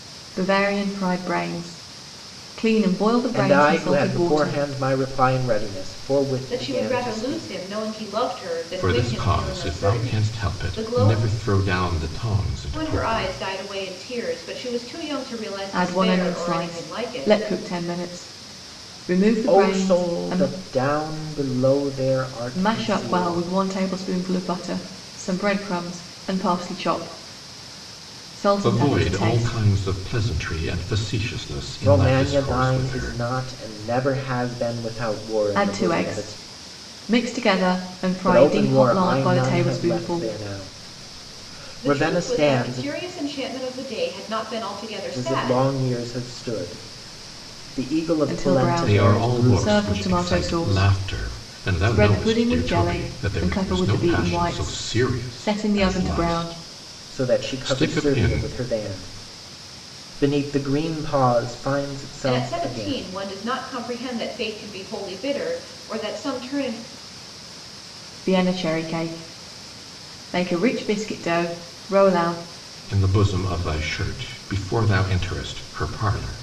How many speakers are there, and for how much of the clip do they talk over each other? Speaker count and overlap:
4, about 34%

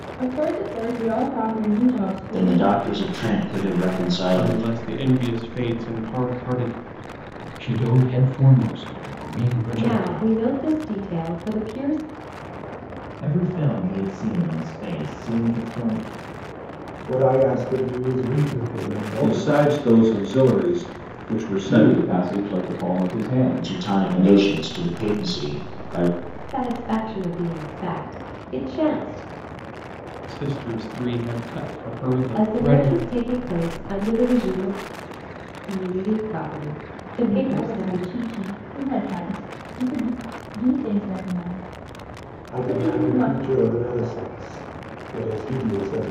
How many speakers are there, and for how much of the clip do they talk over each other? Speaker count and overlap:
9, about 13%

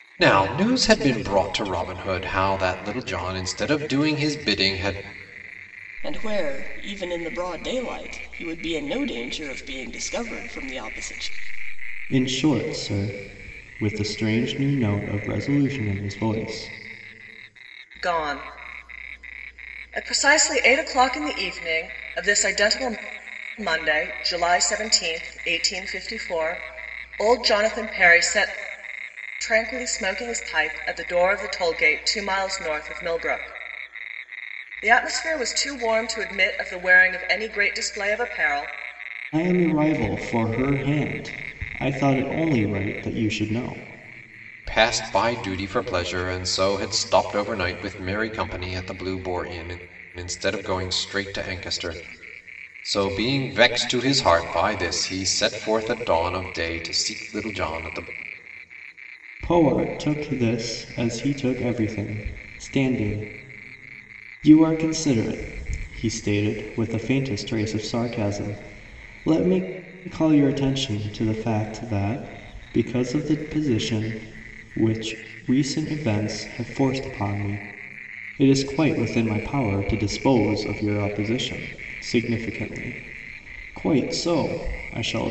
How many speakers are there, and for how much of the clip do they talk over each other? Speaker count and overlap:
4, no overlap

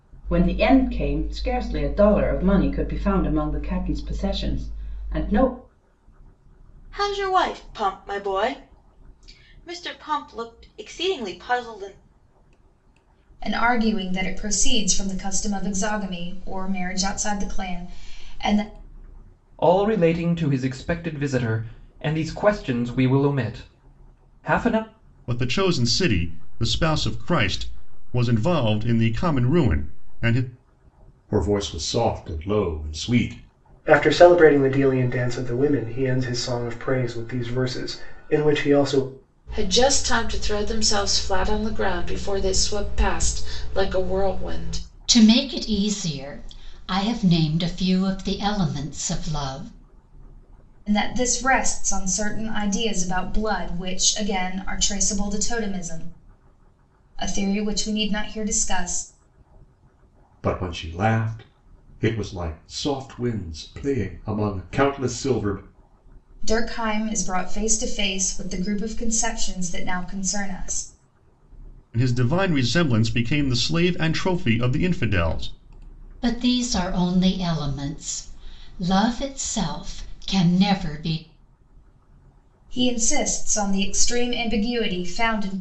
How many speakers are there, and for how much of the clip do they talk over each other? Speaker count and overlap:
9, no overlap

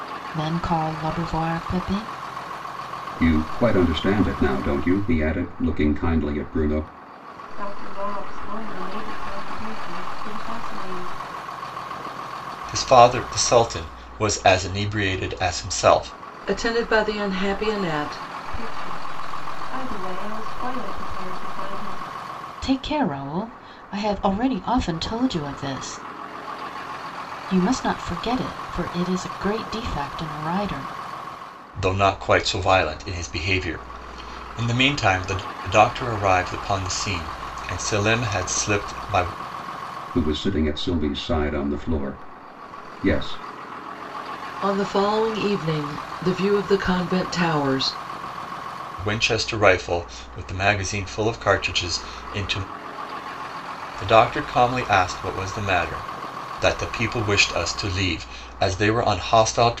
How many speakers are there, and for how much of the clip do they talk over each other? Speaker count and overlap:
5, no overlap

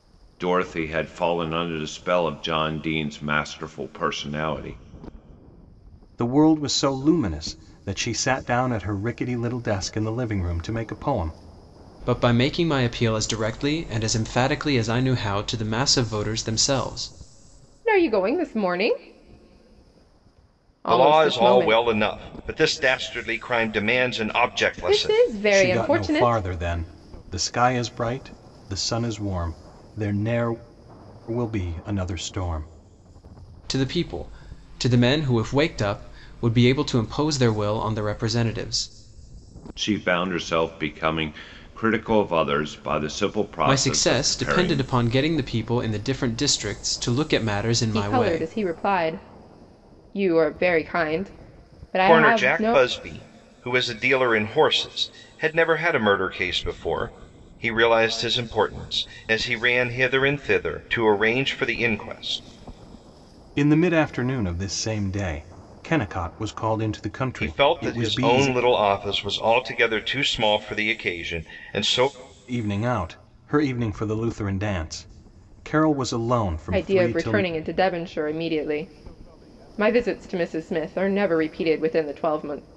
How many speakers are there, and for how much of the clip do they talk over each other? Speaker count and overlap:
5, about 9%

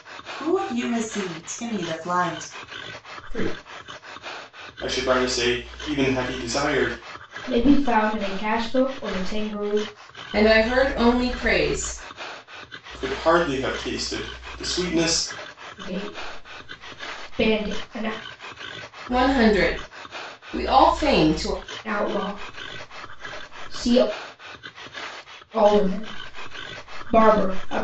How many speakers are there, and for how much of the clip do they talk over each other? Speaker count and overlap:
5, no overlap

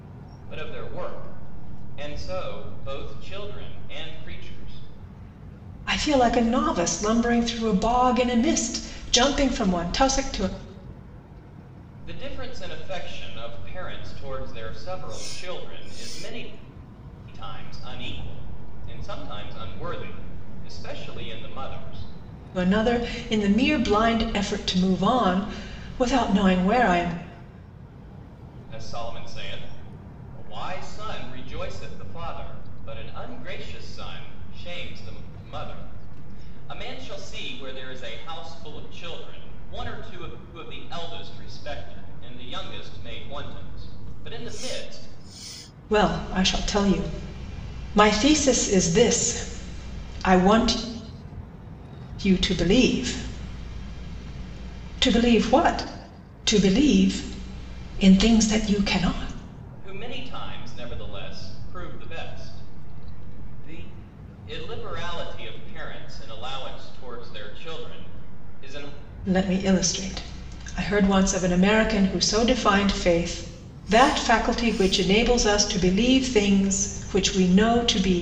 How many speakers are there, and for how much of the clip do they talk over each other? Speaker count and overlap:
2, no overlap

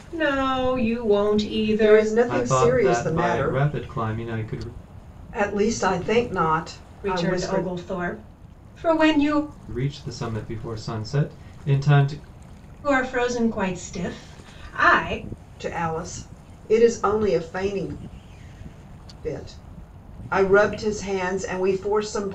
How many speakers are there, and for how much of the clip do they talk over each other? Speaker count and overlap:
3, about 11%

